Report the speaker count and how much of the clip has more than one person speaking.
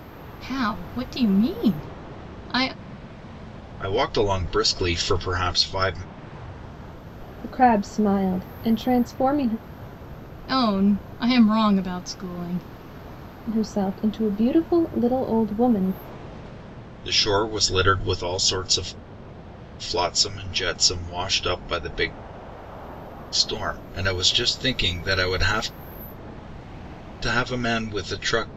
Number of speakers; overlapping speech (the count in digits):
3, no overlap